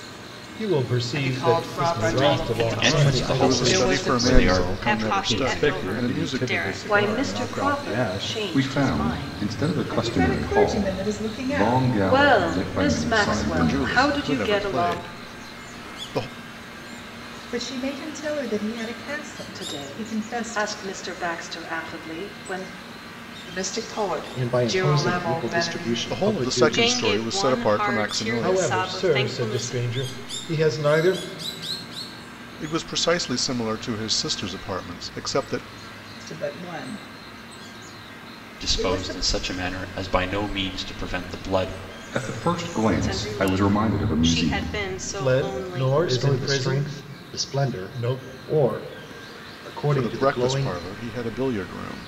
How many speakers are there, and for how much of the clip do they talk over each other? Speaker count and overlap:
ten, about 51%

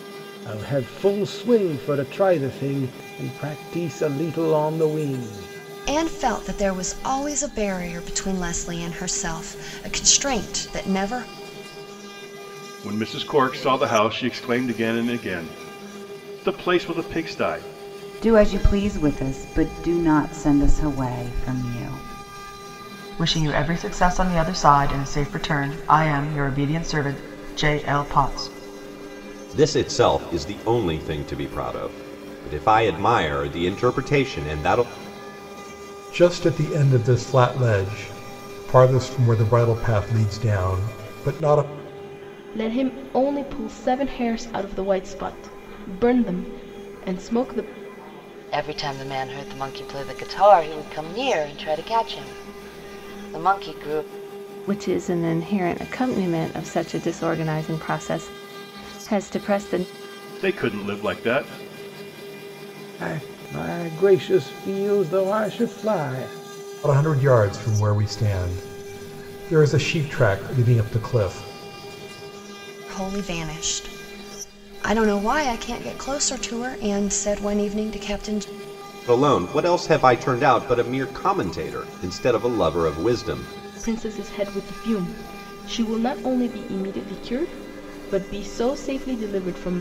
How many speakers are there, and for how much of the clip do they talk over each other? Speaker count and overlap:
ten, no overlap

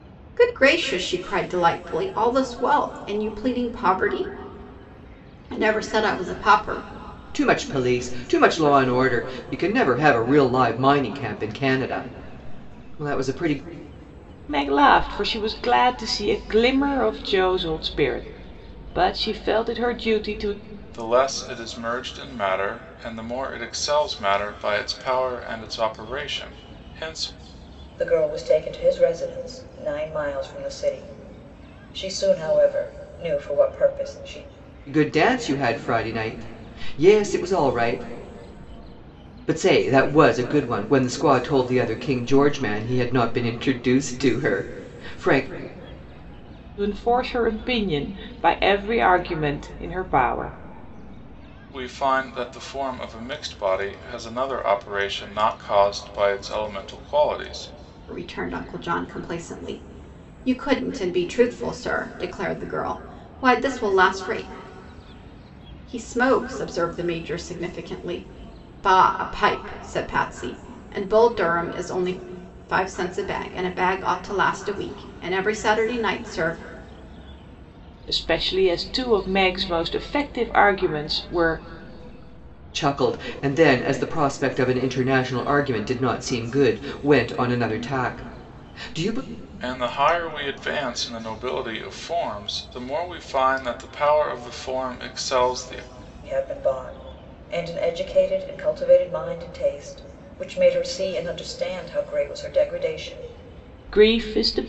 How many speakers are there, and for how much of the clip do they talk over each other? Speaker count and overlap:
five, no overlap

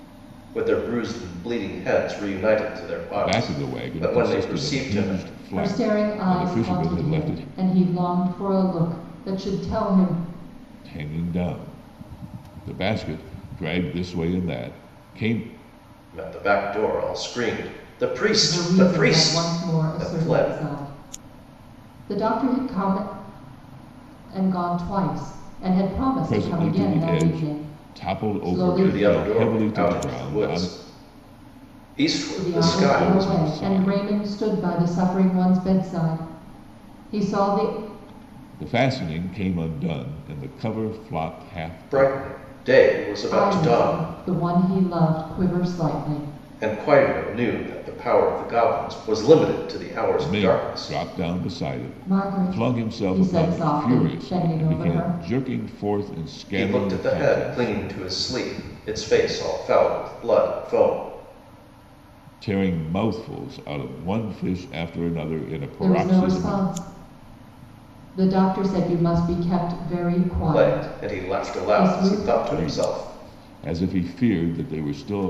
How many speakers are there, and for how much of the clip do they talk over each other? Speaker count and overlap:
three, about 30%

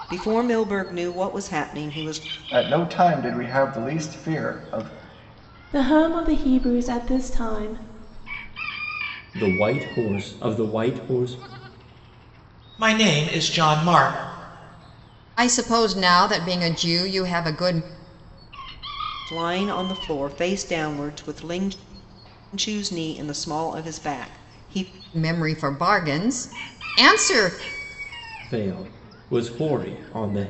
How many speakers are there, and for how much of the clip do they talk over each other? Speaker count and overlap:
six, no overlap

